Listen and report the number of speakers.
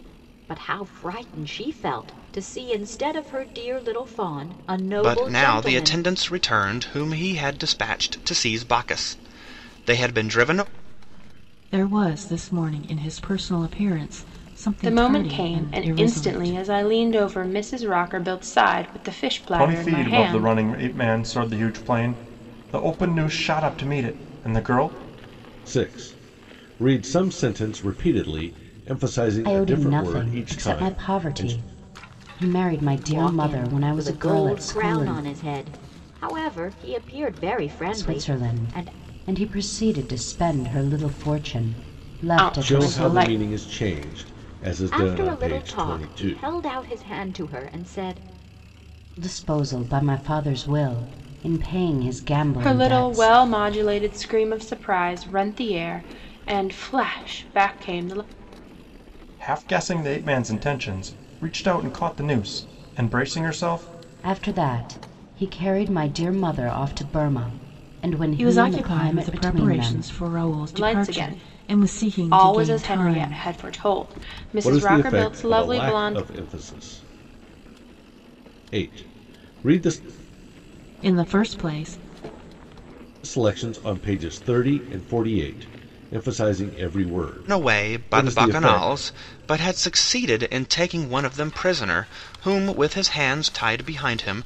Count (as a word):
seven